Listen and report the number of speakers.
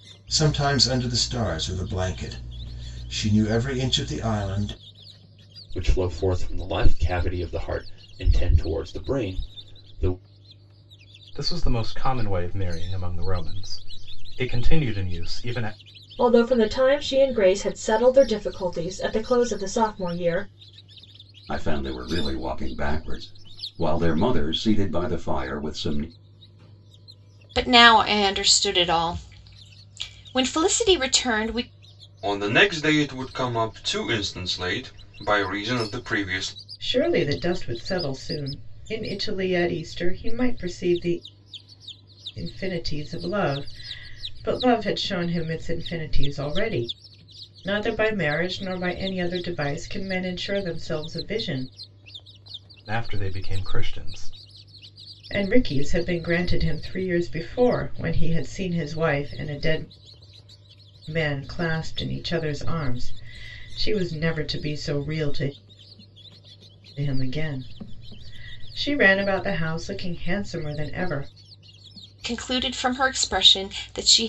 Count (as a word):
eight